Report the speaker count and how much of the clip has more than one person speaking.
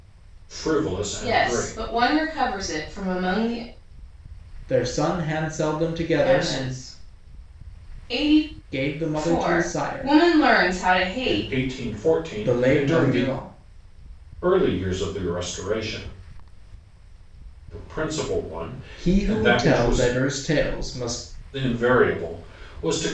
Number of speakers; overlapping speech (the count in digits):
3, about 20%